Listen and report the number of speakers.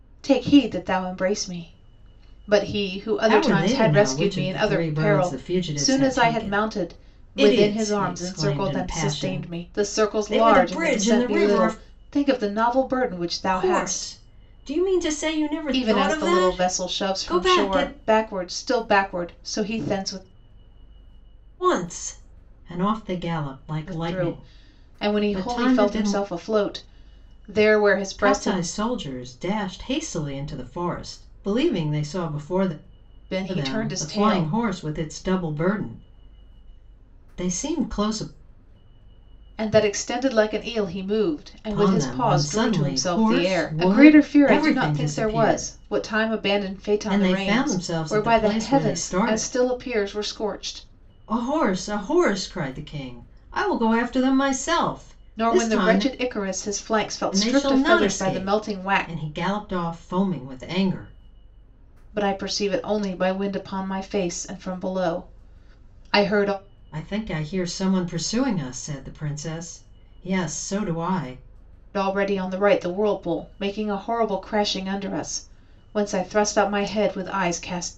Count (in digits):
2